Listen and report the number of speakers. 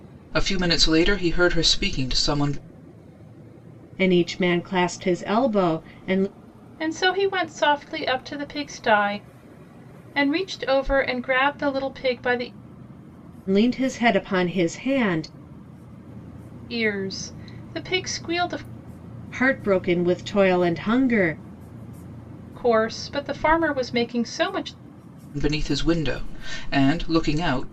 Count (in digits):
3